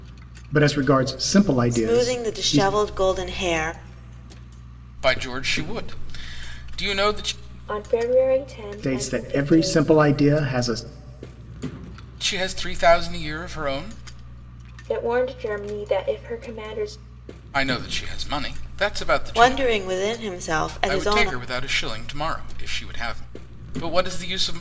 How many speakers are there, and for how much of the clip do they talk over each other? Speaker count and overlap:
4, about 13%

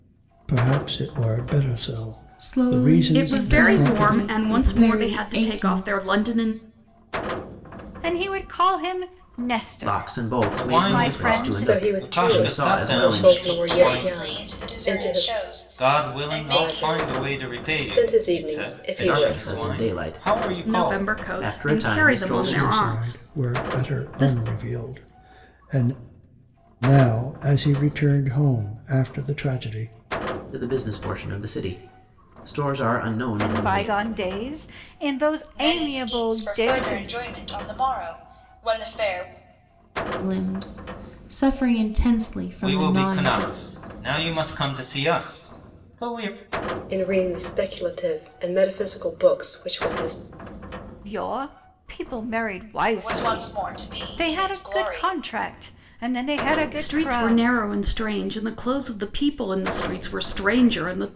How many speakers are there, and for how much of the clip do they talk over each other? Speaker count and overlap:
8, about 39%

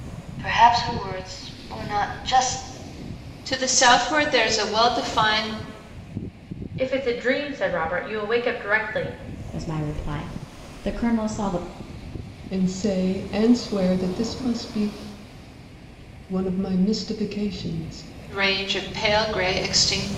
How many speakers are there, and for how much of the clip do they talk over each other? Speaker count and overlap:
5, no overlap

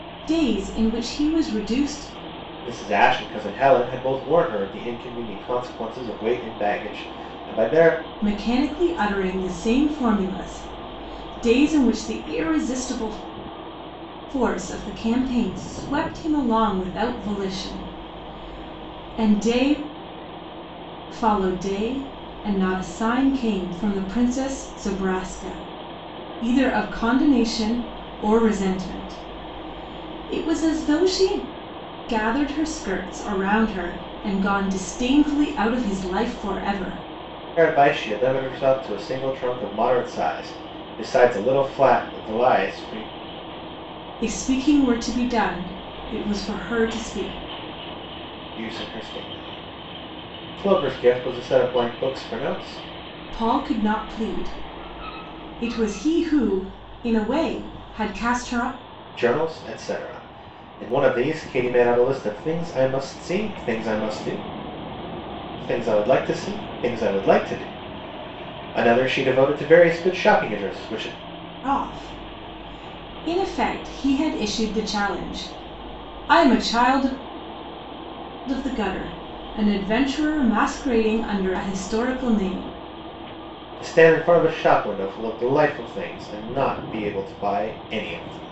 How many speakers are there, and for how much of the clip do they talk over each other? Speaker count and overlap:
2, no overlap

